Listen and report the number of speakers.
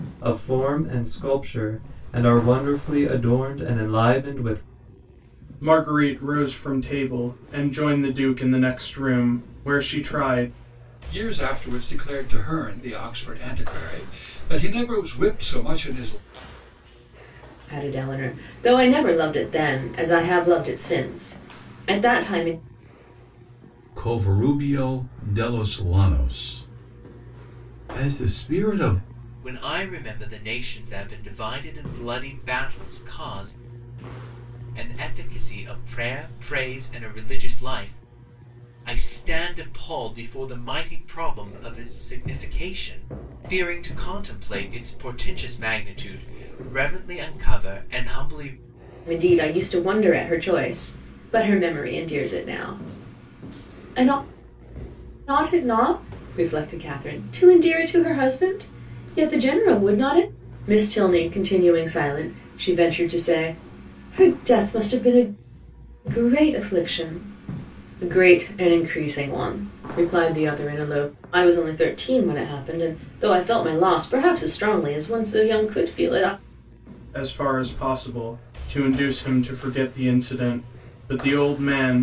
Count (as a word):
six